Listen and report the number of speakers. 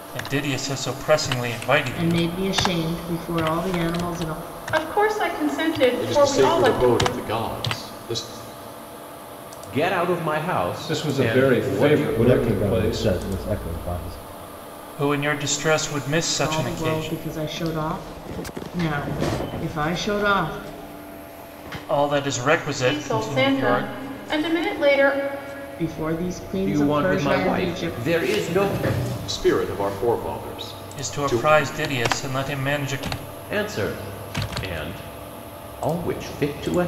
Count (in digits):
7